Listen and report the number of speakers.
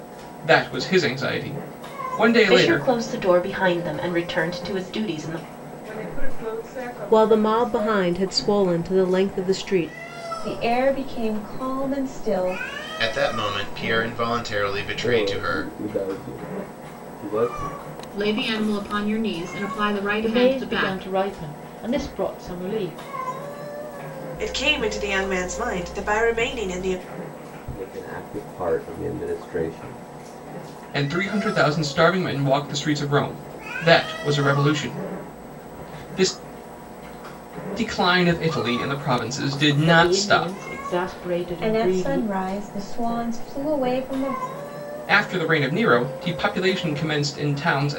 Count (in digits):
10